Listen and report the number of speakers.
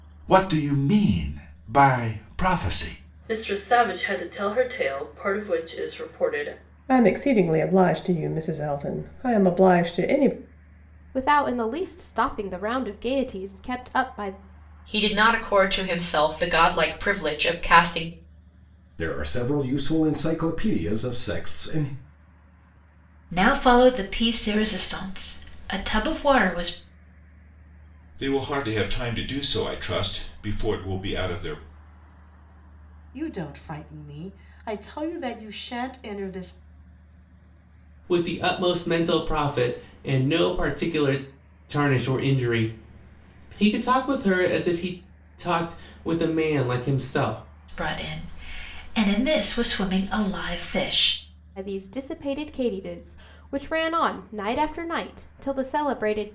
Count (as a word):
ten